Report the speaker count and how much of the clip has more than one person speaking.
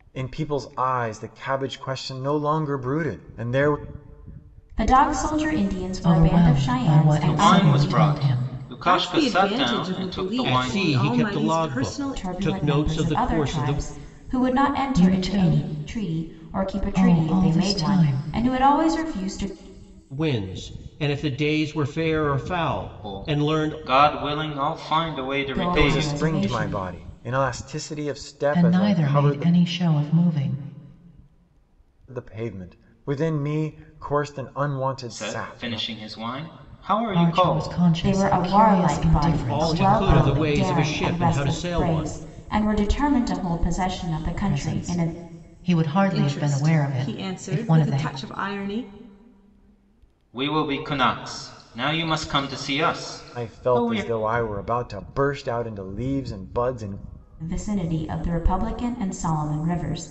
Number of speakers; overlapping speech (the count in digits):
6, about 38%